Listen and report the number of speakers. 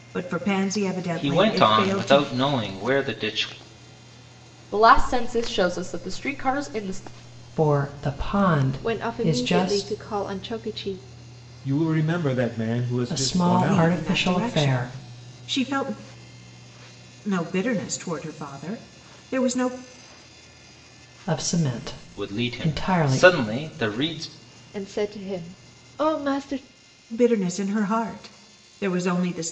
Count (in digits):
6